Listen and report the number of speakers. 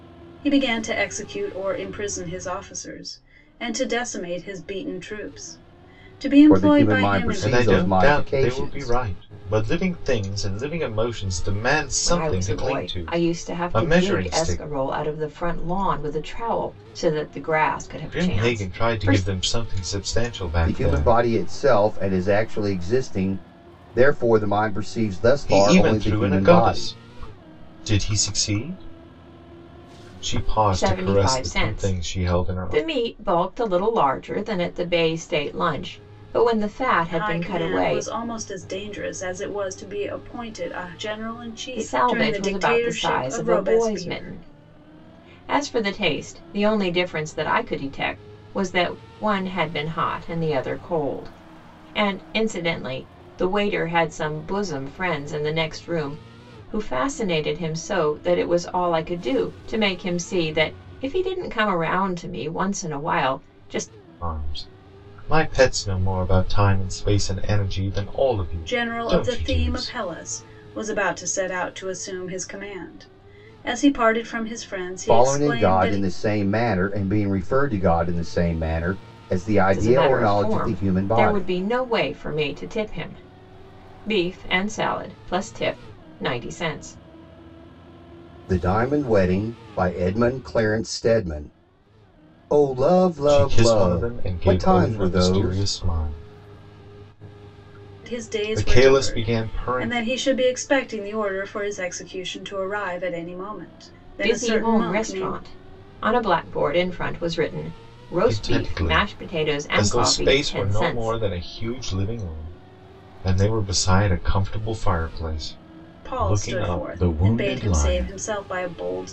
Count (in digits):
4